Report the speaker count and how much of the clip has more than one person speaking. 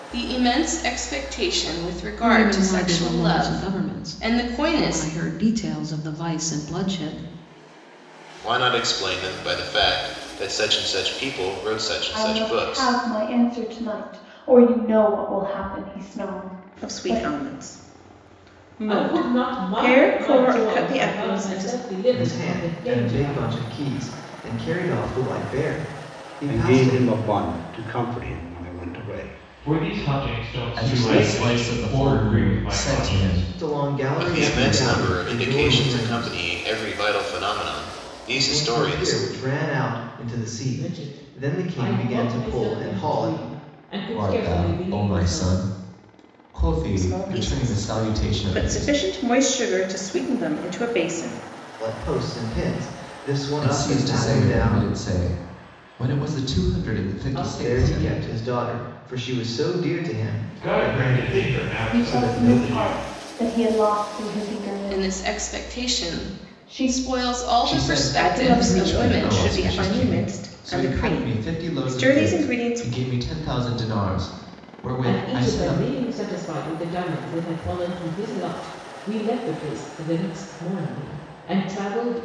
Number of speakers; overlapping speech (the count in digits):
10, about 43%